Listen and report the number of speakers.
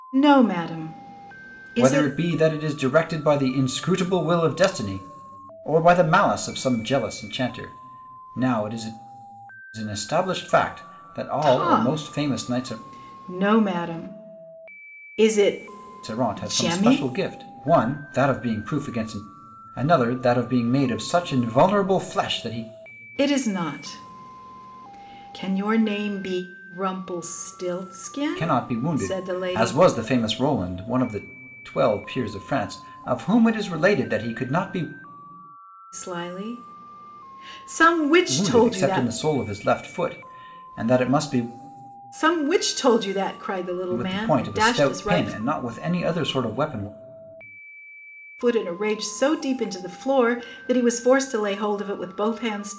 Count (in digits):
2